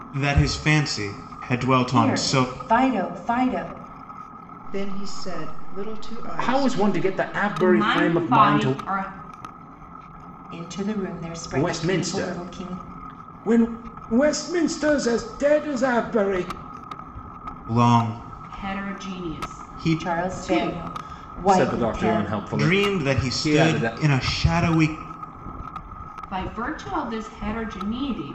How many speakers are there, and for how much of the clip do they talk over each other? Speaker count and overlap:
five, about 30%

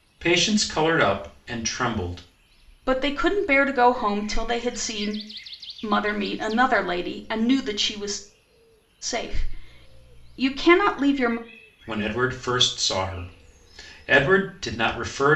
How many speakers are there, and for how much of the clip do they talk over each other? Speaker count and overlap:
two, no overlap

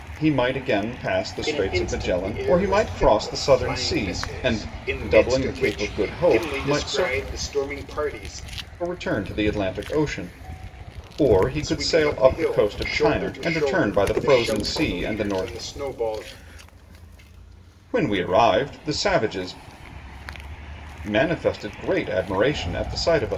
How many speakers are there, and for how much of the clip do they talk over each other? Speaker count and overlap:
two, about 39%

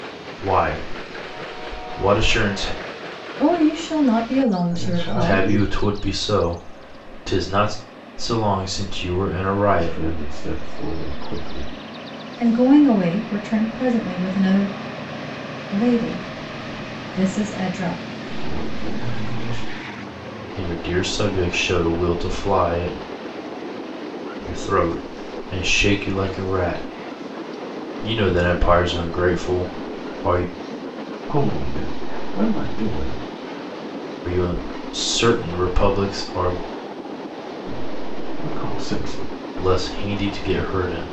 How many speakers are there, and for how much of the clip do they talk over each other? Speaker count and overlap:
three, about 3%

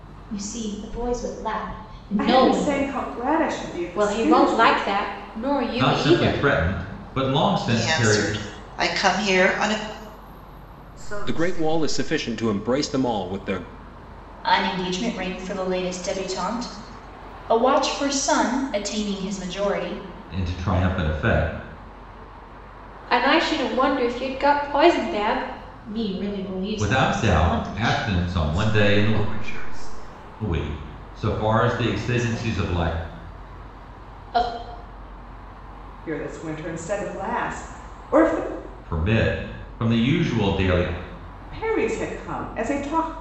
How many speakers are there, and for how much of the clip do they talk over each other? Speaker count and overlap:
eight, about 16%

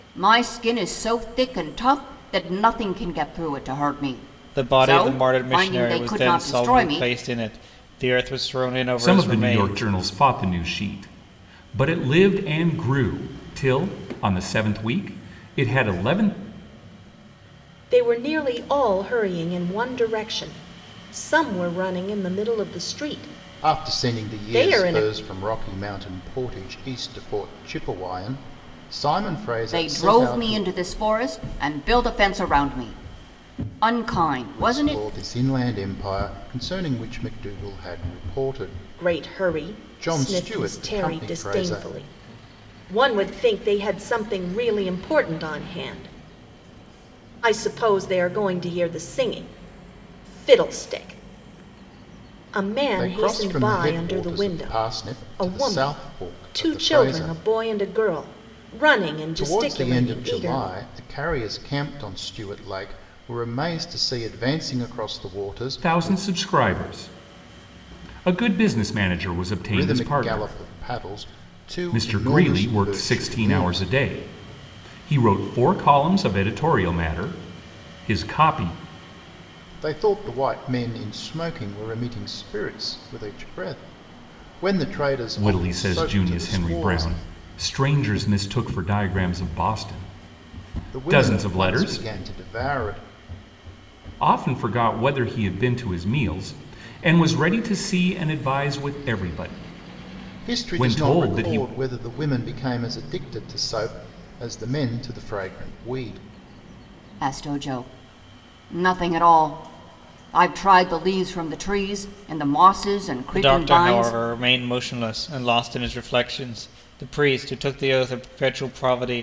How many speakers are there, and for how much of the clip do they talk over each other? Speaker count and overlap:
five, about 20%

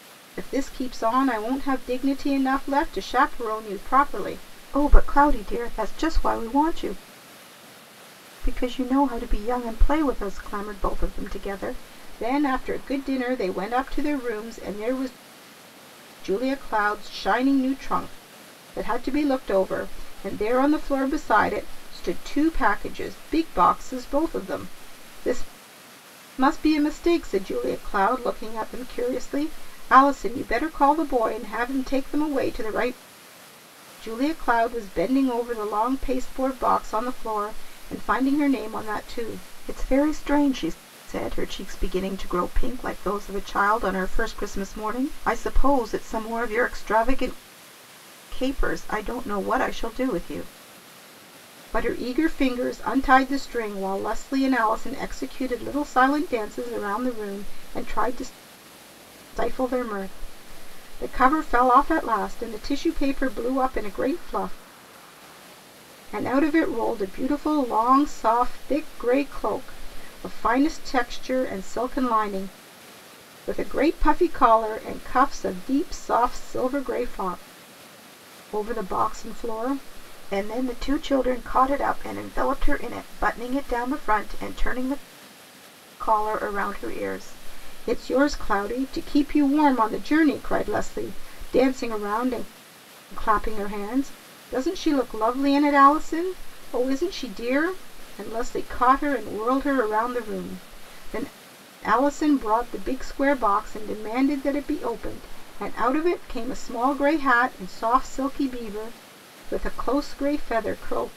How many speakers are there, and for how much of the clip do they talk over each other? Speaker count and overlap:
one, no overlap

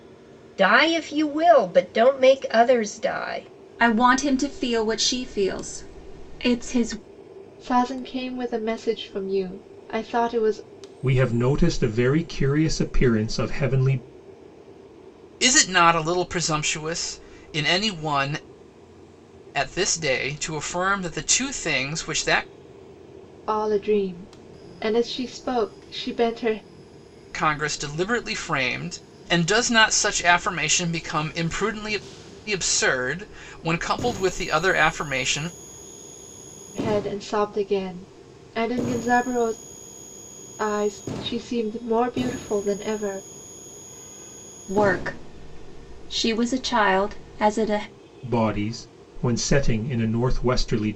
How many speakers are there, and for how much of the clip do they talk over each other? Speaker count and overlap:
five, no overlap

